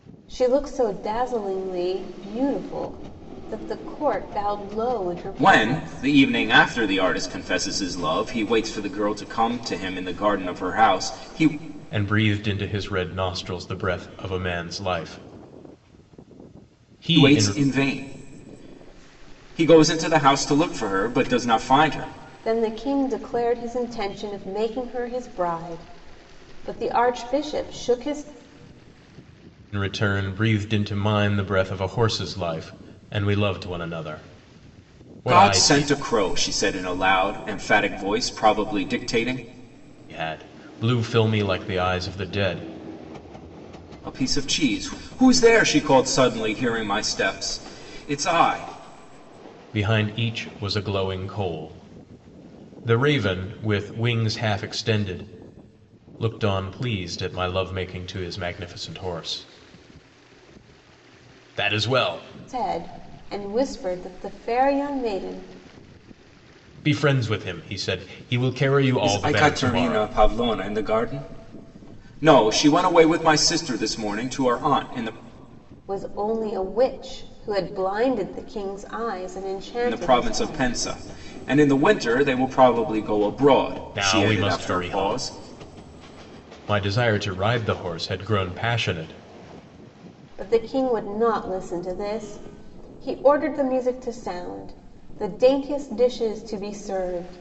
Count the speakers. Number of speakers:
3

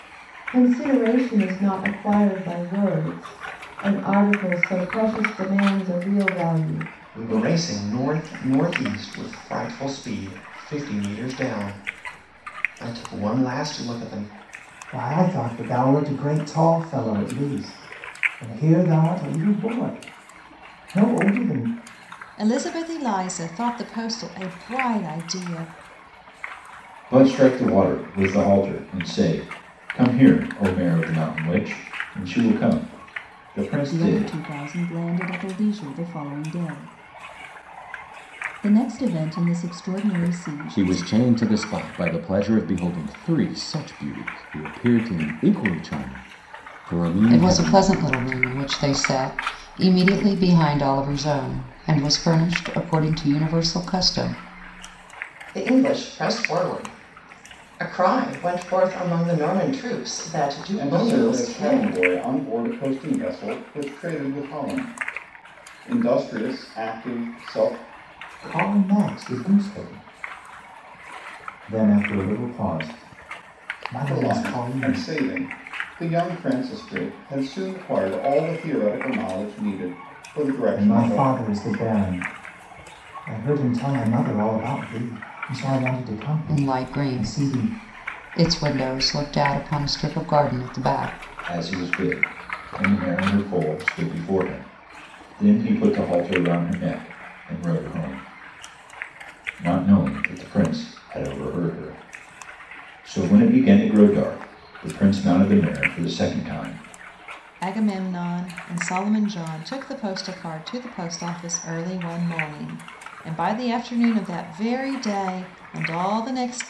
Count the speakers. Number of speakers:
10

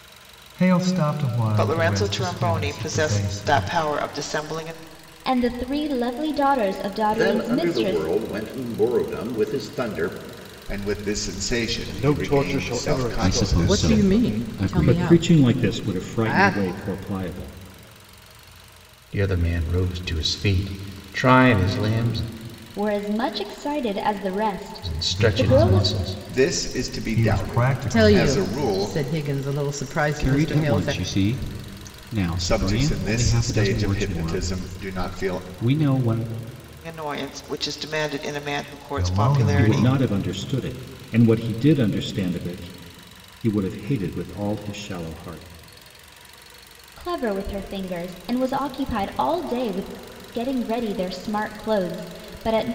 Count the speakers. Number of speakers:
10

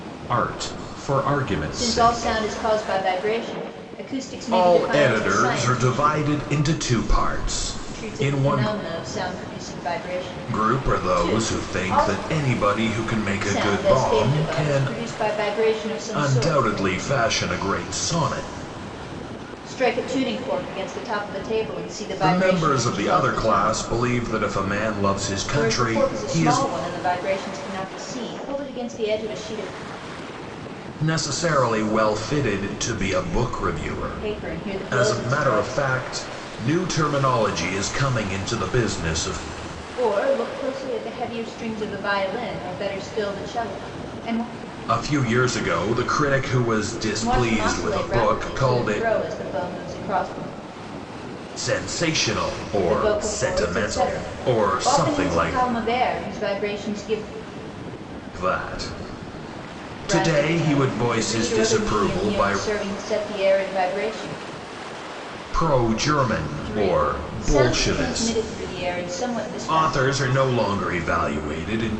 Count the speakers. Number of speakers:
2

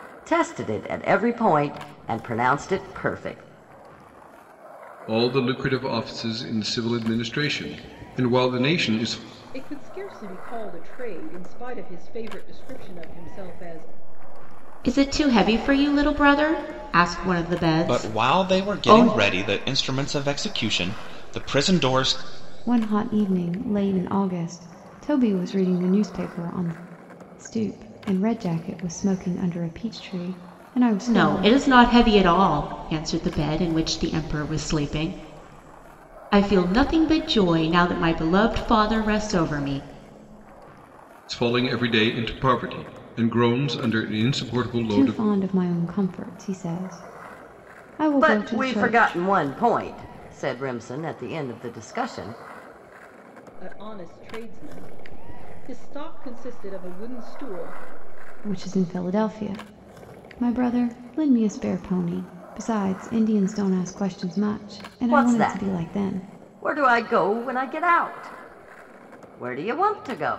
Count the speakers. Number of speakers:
6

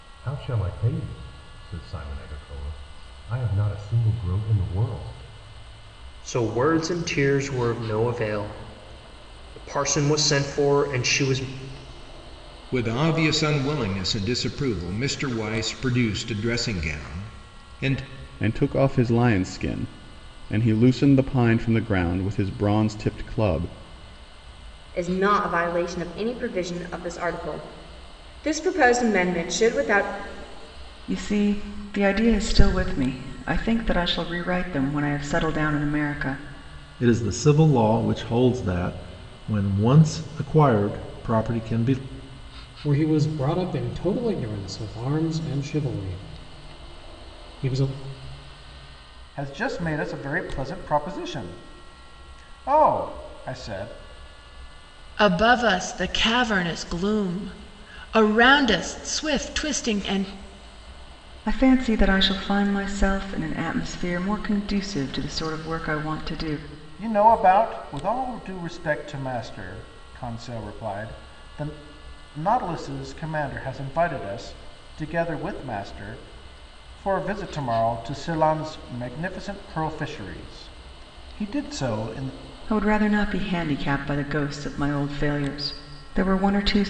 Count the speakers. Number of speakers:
10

